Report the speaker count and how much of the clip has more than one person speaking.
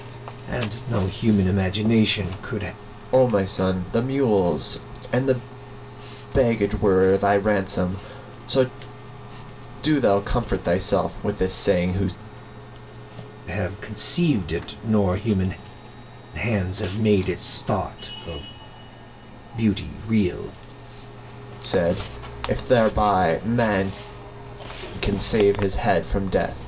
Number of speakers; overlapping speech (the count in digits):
2, no overlap